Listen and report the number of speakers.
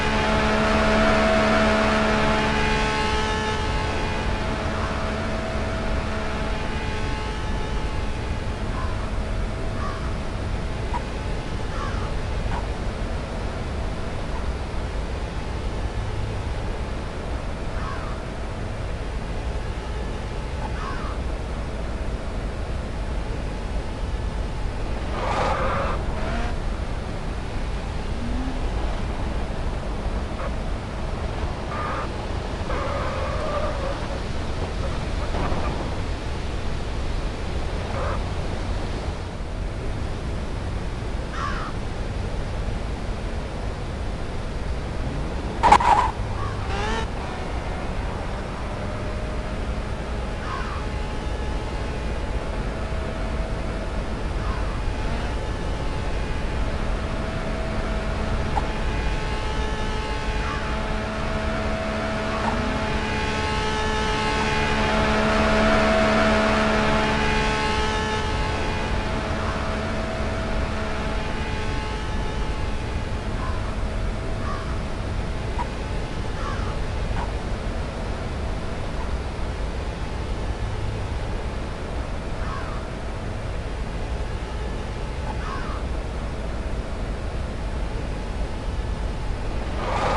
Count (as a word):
zero